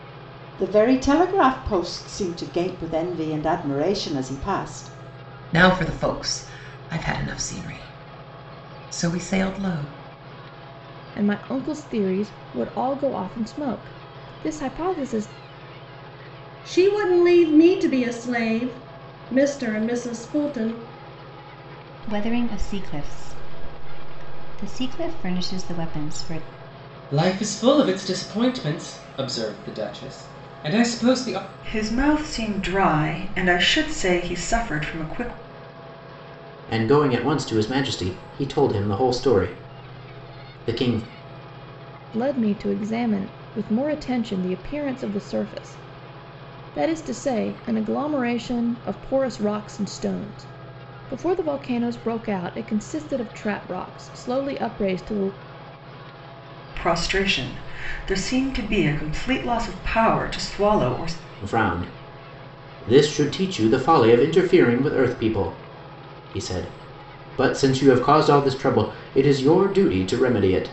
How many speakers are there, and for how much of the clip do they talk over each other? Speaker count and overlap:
eight, no overlap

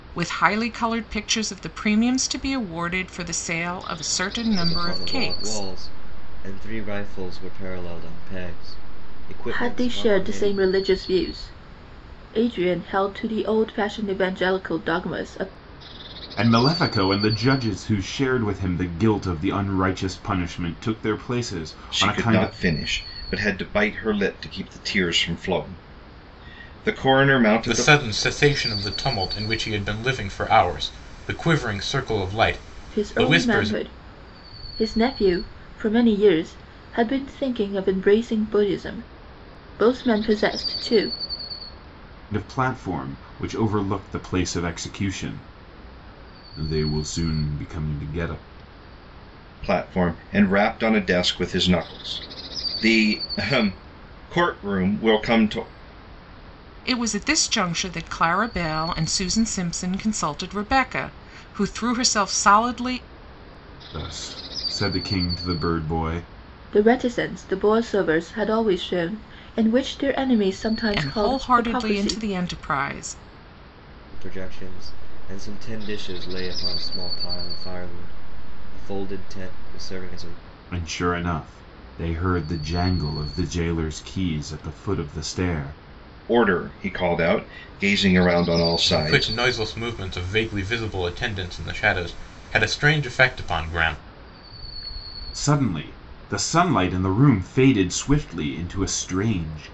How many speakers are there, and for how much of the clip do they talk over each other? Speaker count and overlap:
six, about 6%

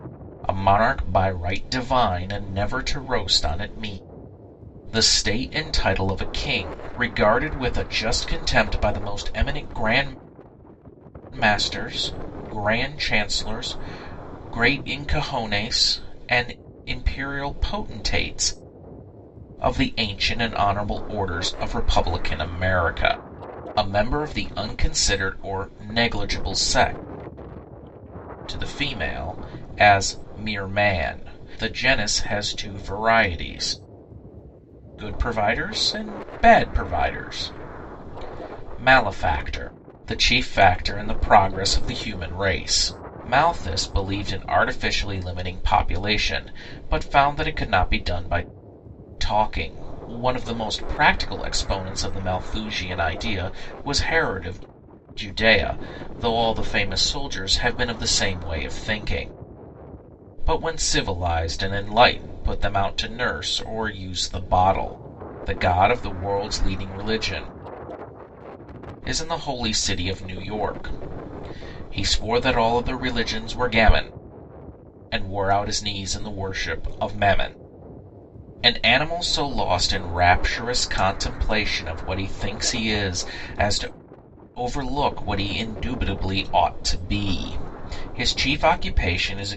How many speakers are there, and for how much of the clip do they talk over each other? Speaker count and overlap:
one, no overlap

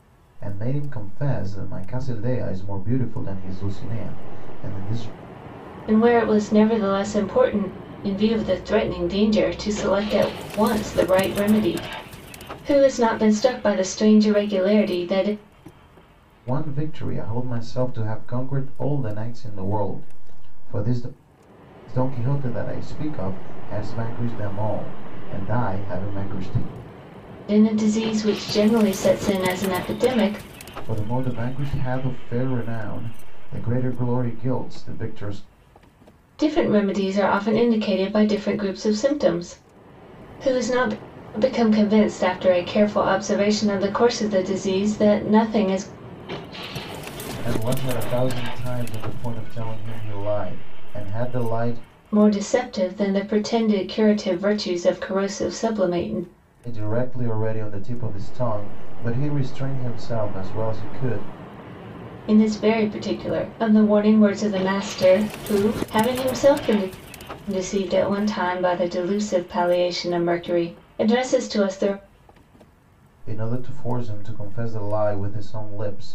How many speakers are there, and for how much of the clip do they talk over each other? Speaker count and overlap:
two, no overlap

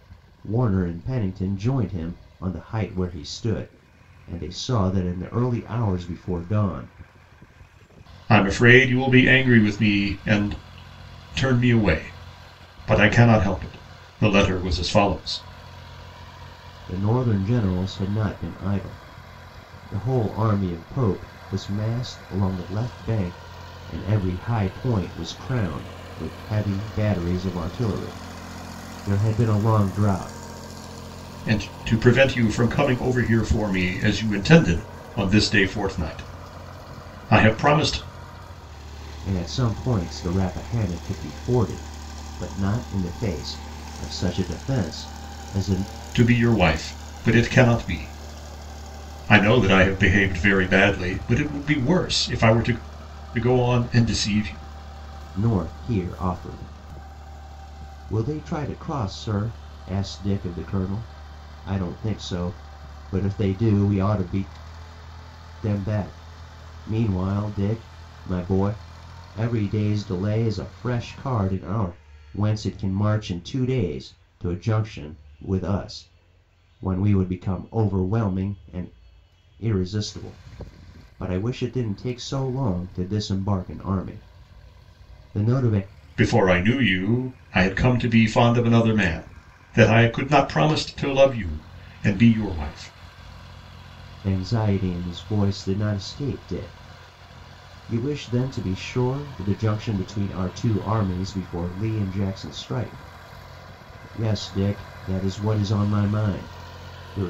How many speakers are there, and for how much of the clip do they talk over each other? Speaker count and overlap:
two, no overlap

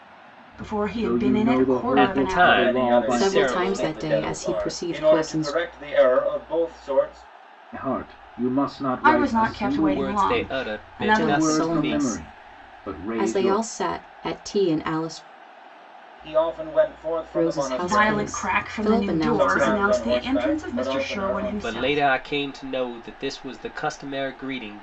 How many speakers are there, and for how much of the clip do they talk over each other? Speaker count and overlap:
five, about 53%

